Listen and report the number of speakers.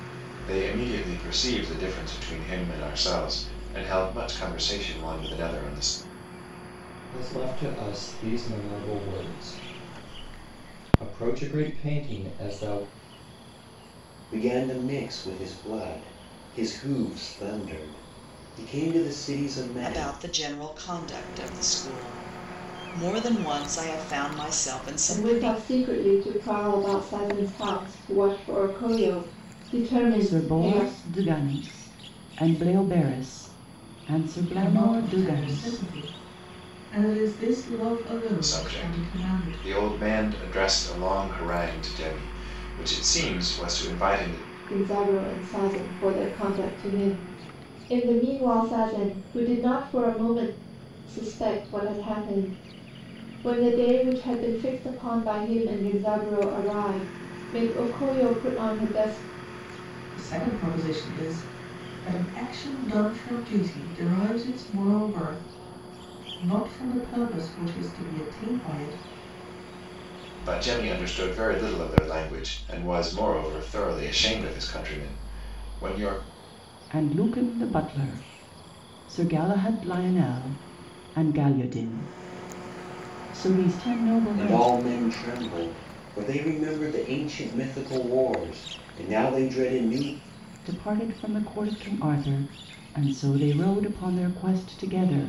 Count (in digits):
7